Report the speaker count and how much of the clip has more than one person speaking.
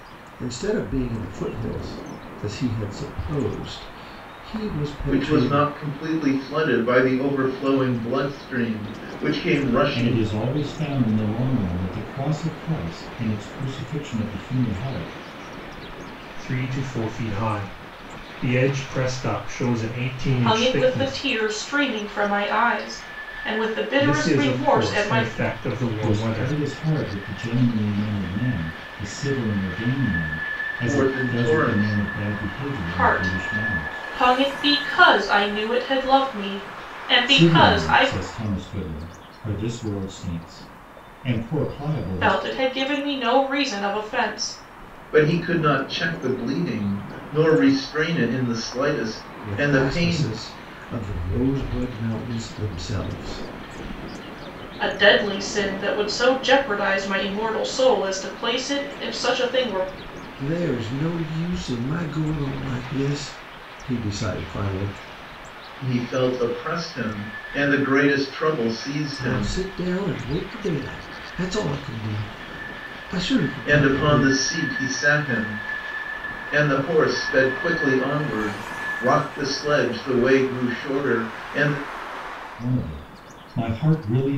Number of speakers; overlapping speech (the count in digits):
5, about 11%